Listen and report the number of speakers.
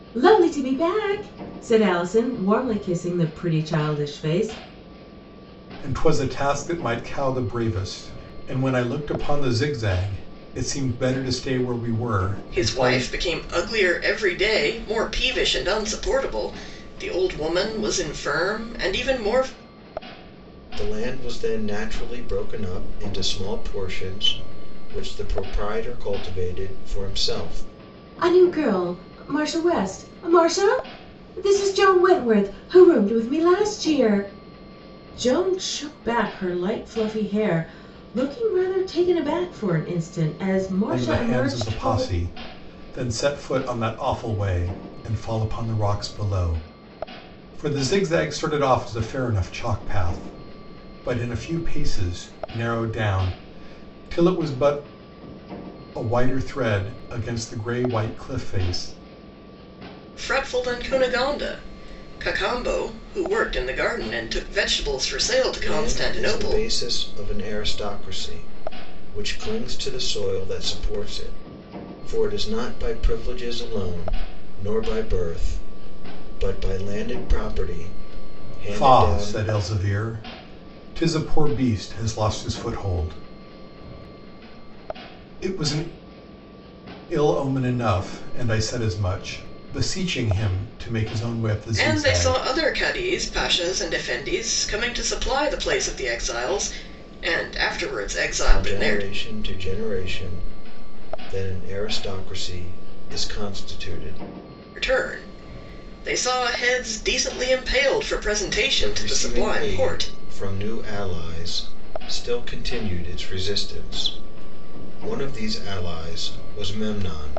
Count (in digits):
4